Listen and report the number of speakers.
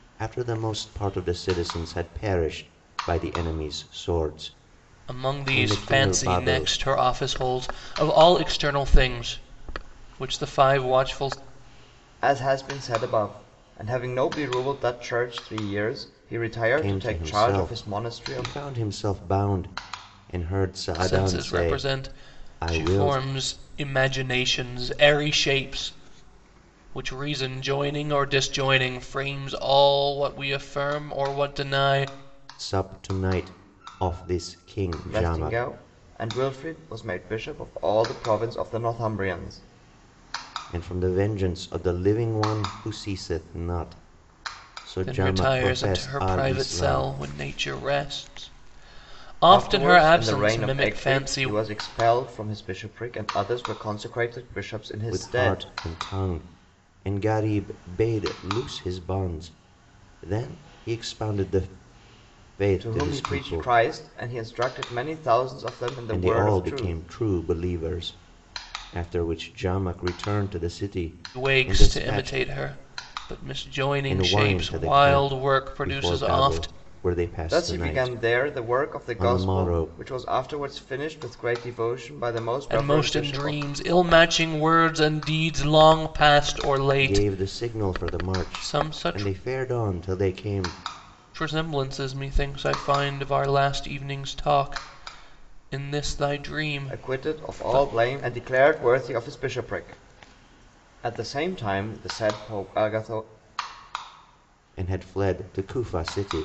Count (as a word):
three